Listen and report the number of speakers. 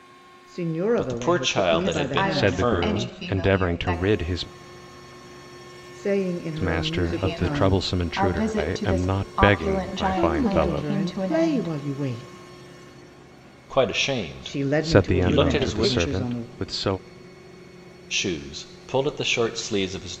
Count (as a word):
four